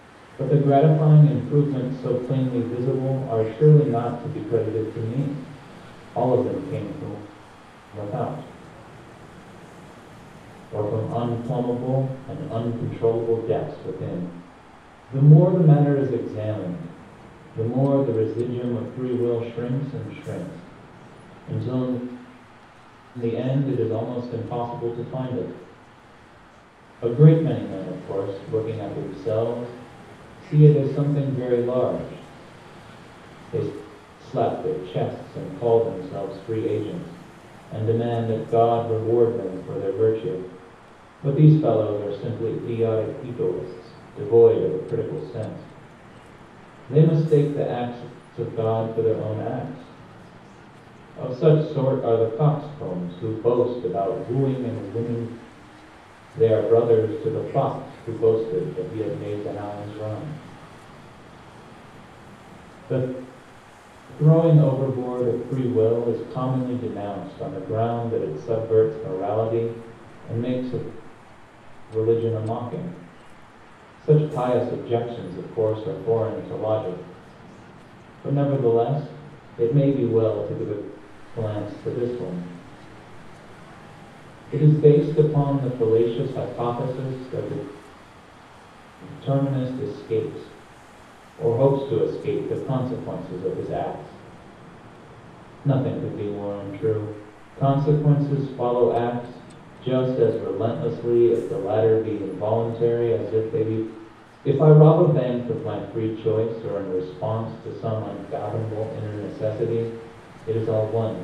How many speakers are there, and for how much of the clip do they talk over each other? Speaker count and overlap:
1, no overlap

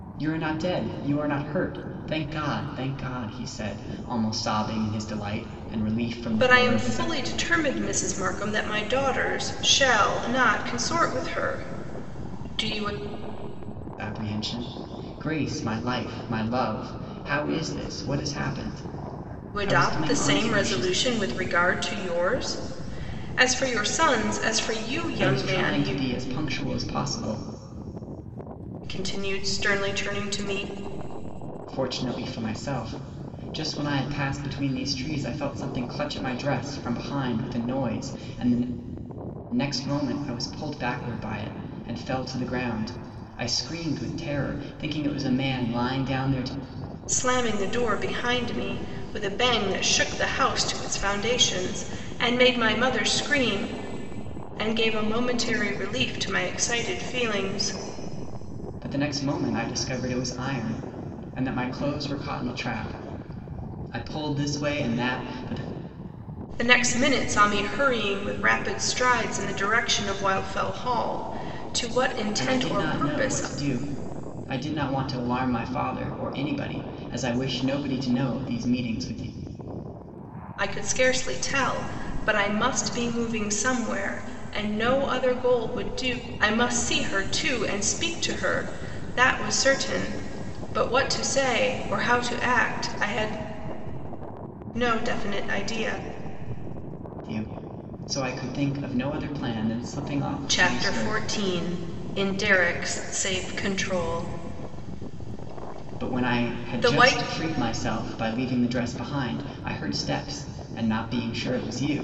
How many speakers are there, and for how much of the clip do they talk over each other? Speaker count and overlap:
2, about 6%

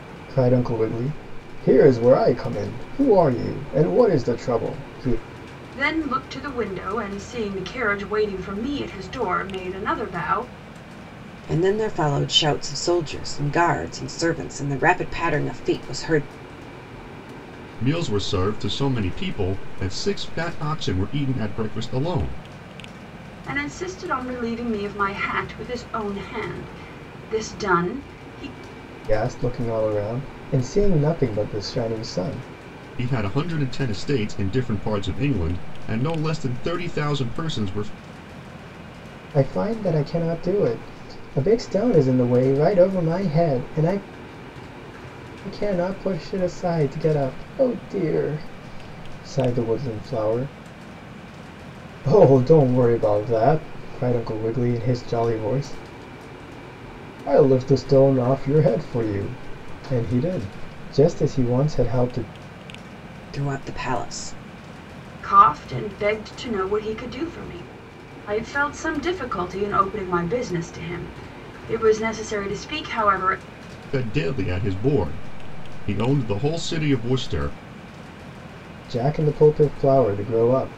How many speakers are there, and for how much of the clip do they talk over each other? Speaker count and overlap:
4, no overlap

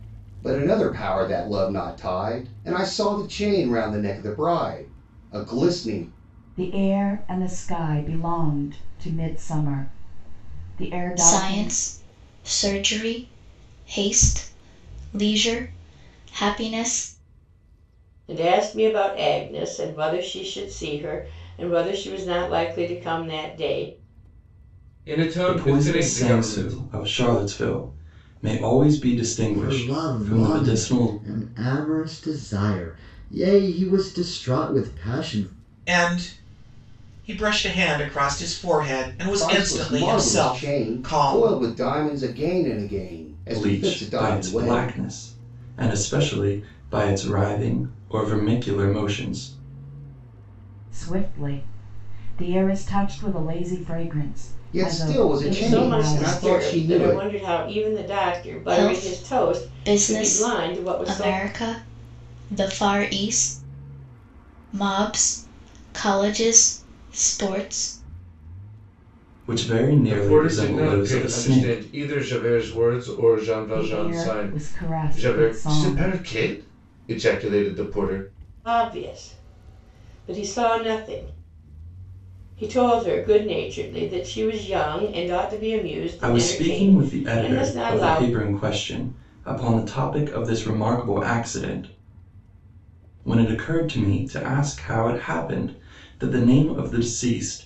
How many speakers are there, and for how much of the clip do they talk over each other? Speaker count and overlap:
8, about 19%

